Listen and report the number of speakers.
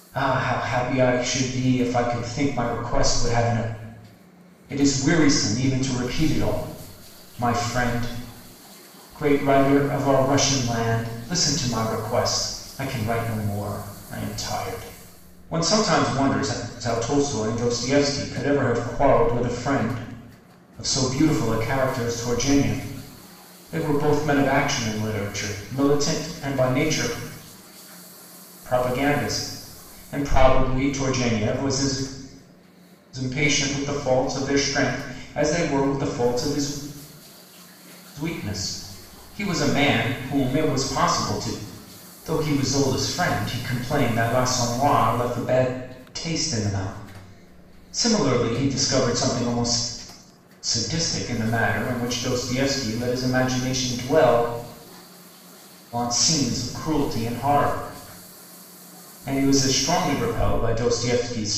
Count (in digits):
1